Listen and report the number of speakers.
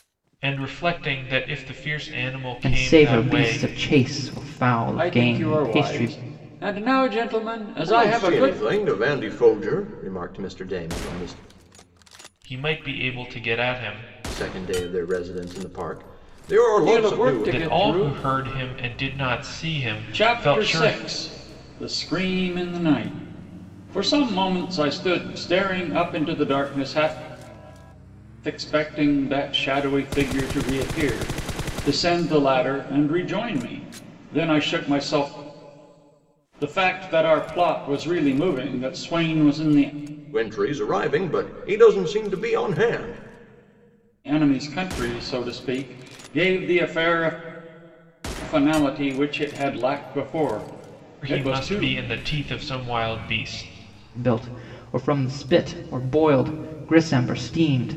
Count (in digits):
4